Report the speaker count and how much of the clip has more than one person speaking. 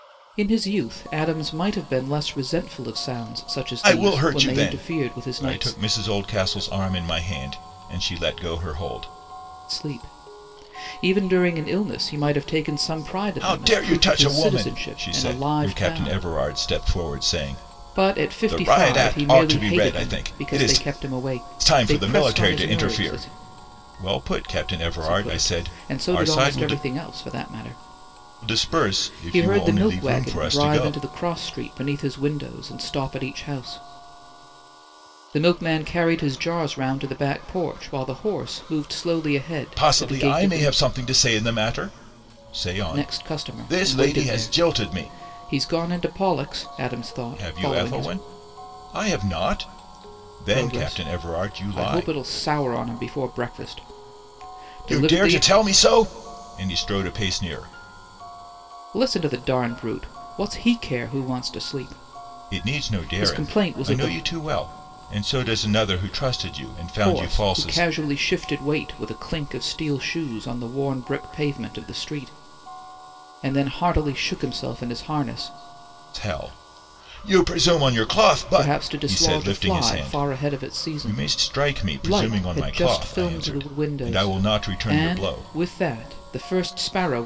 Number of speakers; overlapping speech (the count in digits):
2, about 34%